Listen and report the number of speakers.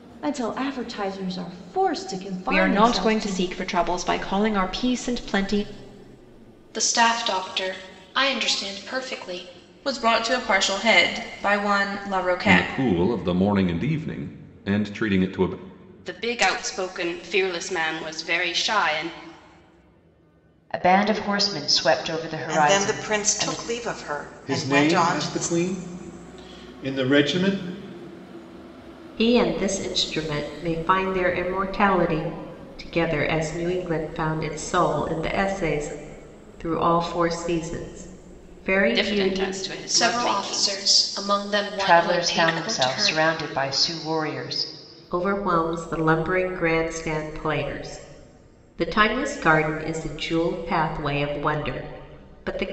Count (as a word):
ten